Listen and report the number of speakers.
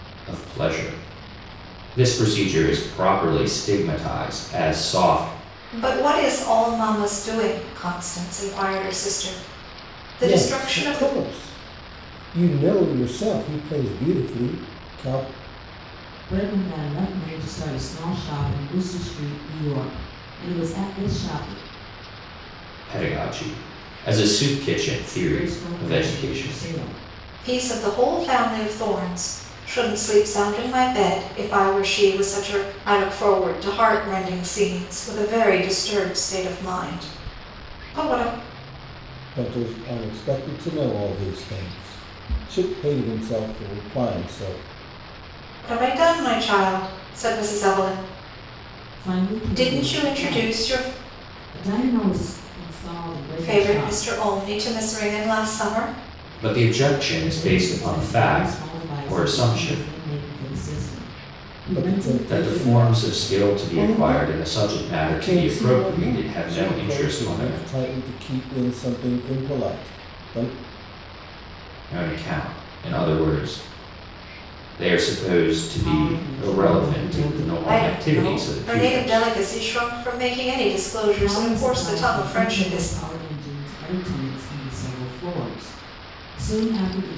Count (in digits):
4